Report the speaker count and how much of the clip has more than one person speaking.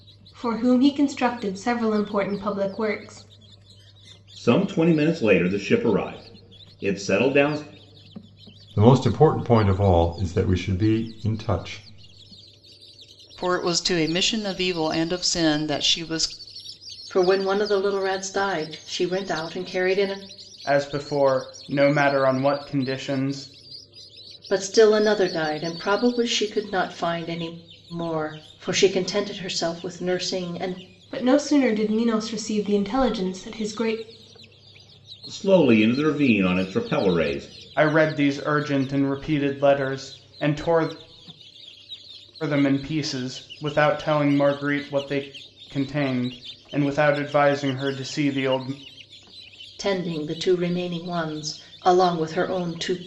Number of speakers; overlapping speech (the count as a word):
six, no overlap